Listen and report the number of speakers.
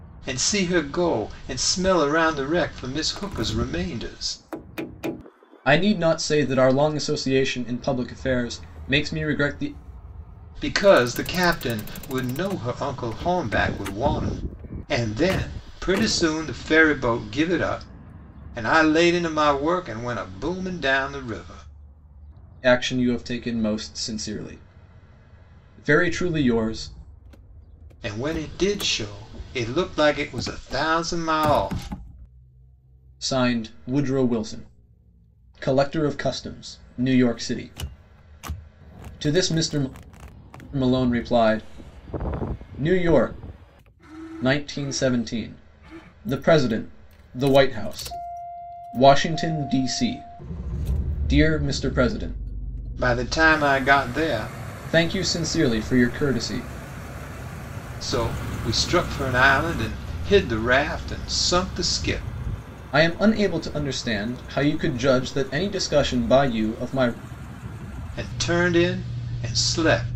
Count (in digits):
2